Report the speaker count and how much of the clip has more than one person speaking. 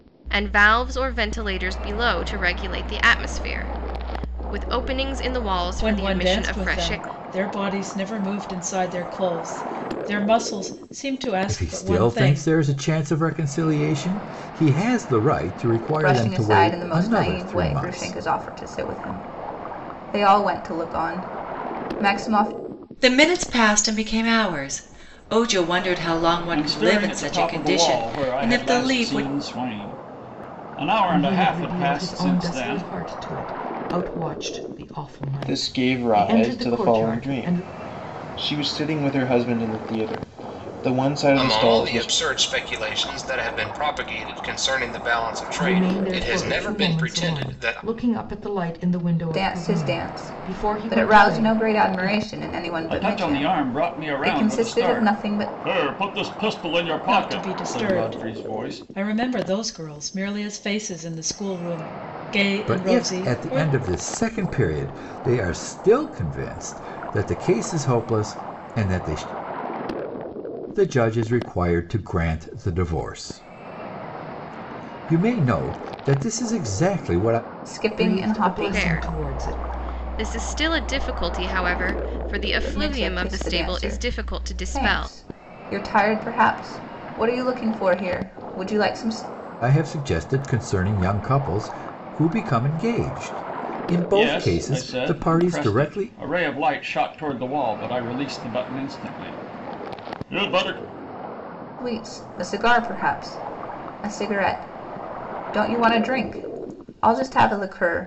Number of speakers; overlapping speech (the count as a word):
nine, about 27%